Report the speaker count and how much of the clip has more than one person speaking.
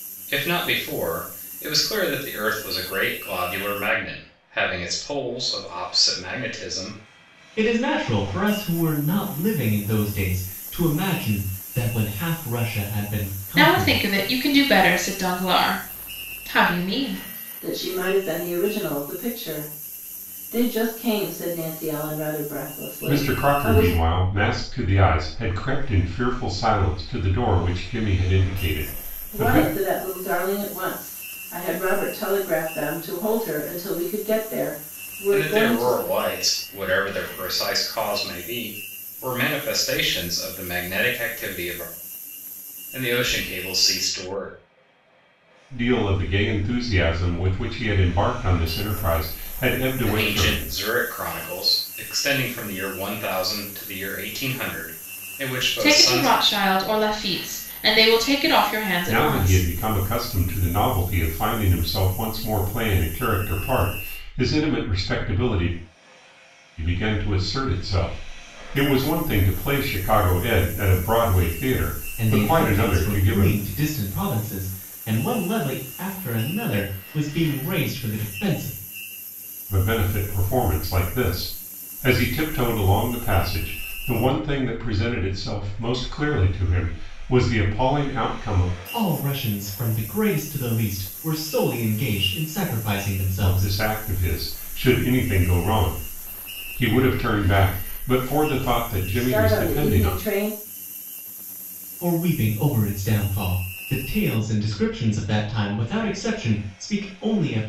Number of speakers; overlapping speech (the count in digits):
5, about 7%